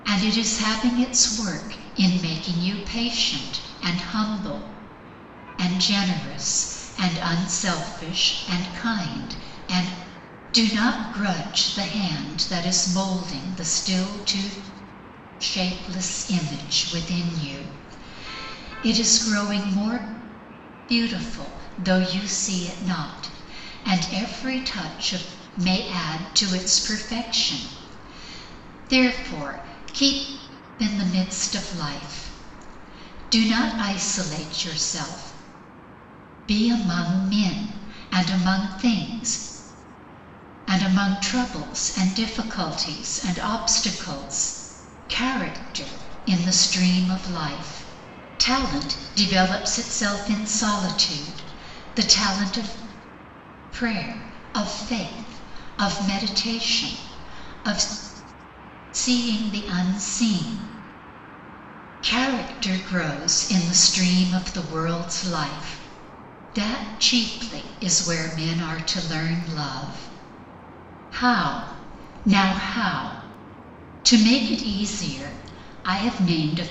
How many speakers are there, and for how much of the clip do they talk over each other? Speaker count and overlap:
one, no overlap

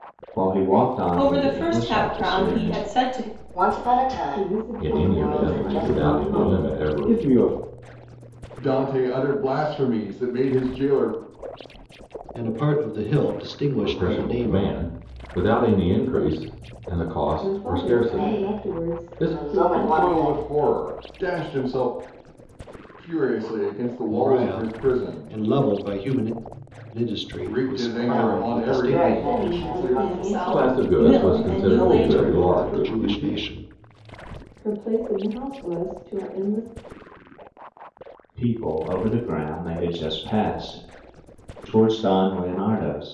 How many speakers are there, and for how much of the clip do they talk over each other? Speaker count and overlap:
eight, about 37%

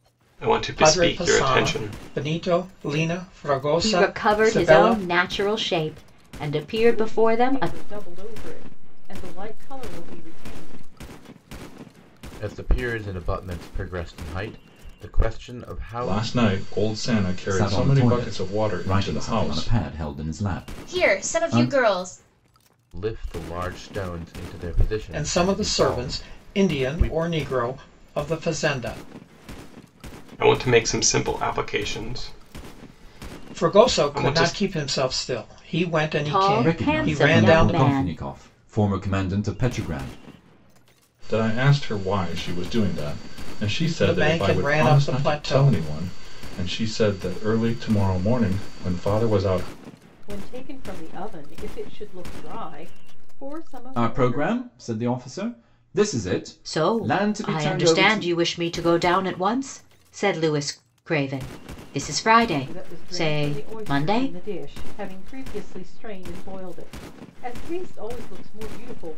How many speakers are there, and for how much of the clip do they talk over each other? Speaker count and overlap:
eight, about 26%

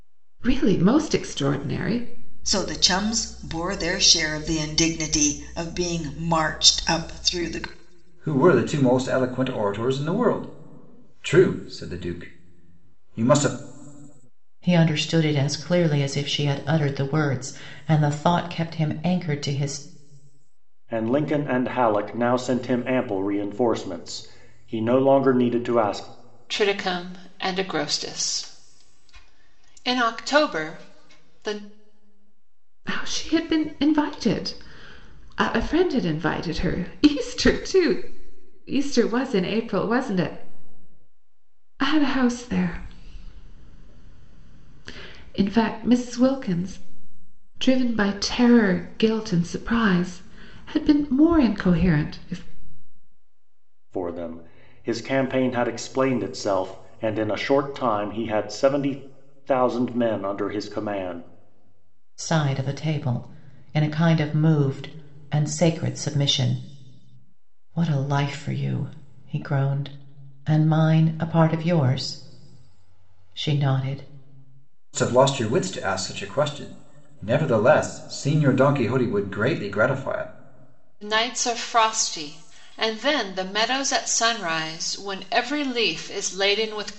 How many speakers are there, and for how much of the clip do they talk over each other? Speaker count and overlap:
six, no overlap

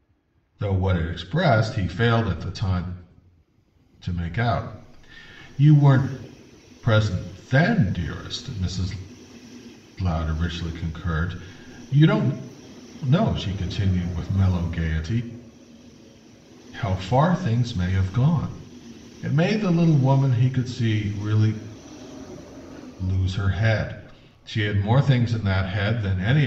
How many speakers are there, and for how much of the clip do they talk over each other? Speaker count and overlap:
one, no overlap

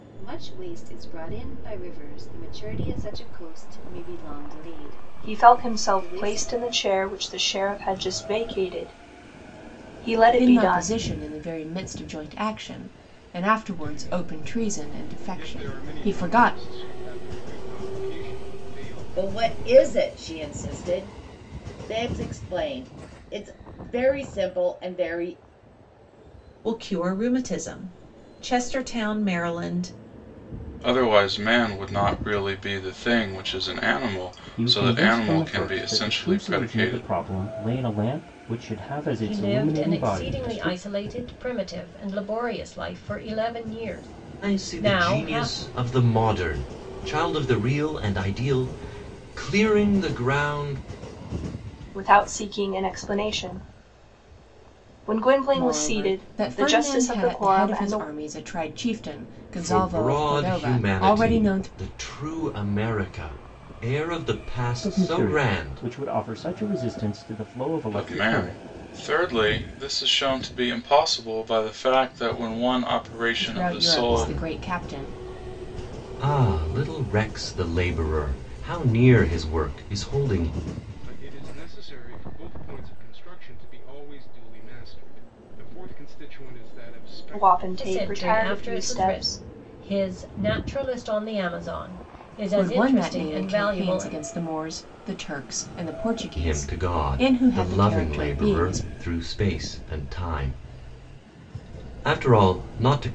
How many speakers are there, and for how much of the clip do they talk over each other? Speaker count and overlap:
ten, about 25%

